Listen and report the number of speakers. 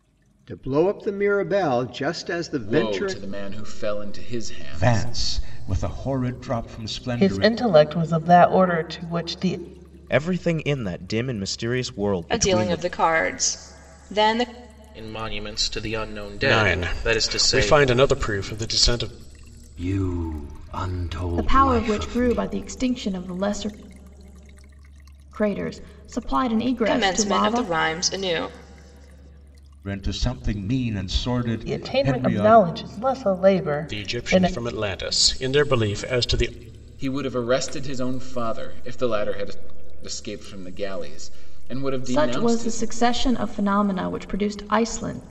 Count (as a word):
ten